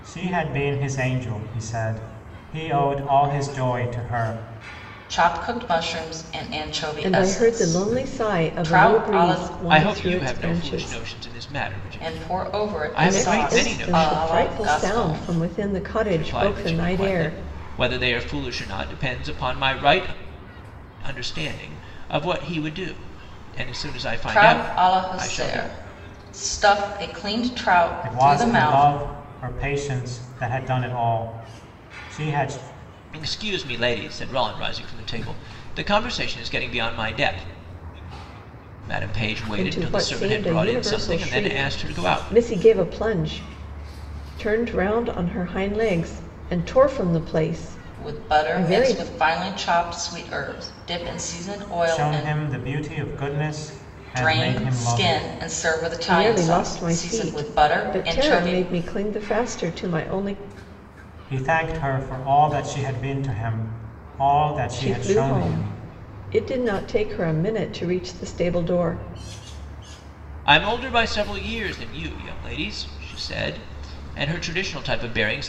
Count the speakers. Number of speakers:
4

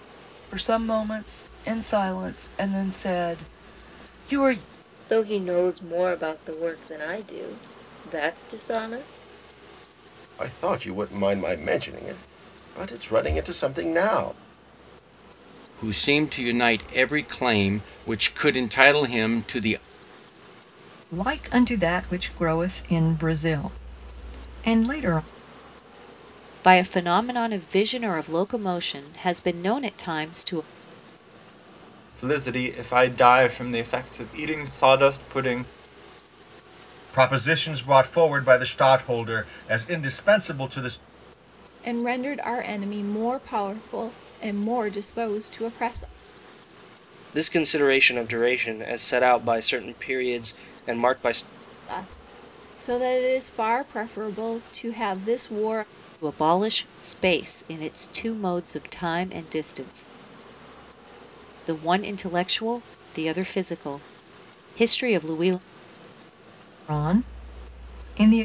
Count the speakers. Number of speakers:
10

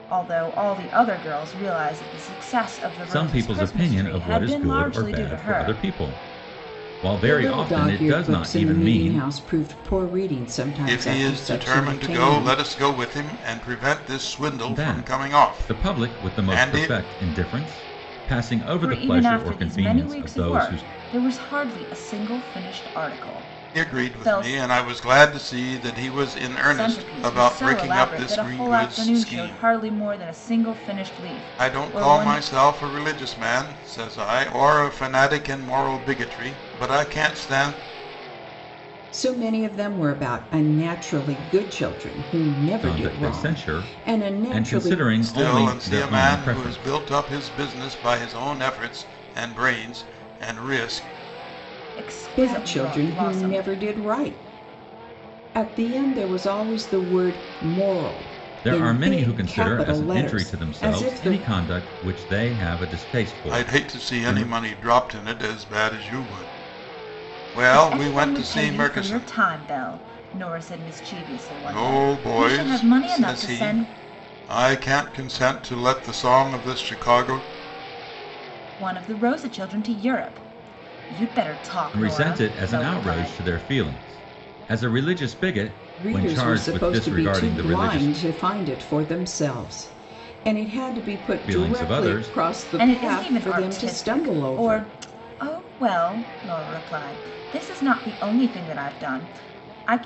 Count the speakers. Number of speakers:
4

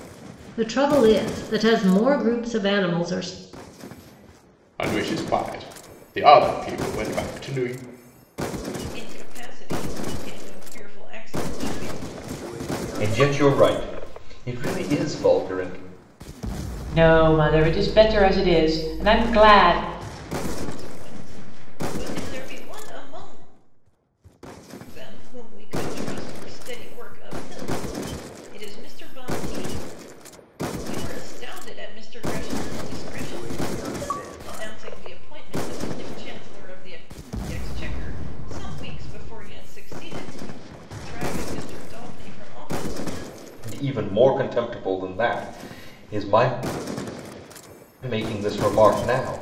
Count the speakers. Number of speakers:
5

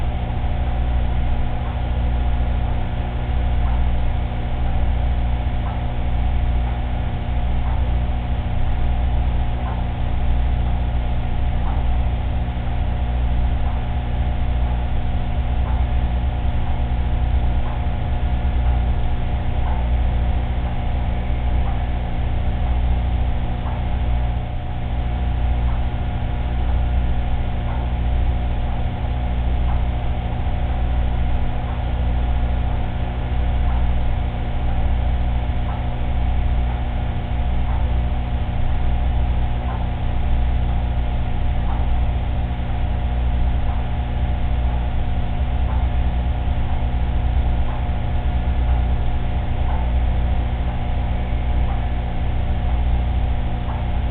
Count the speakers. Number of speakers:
0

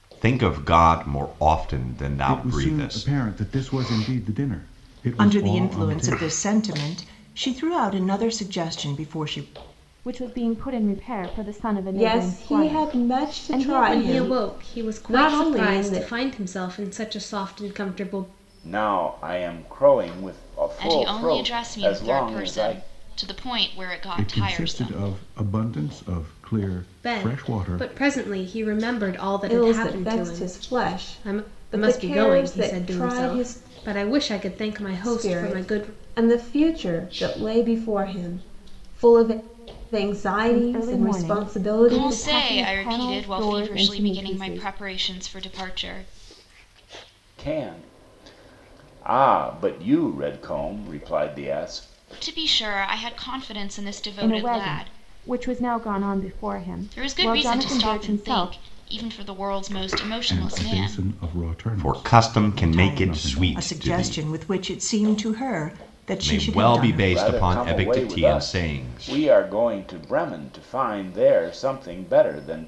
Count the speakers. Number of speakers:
8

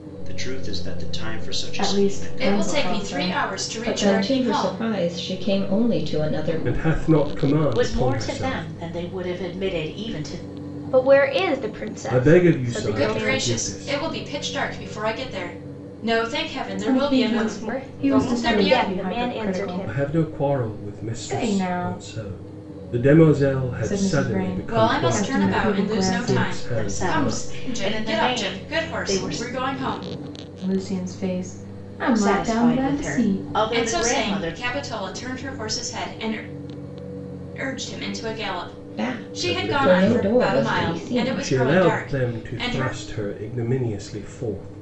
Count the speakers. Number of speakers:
8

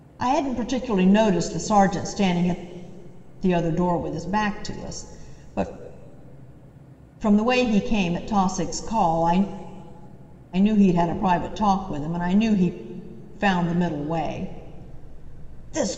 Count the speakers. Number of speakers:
1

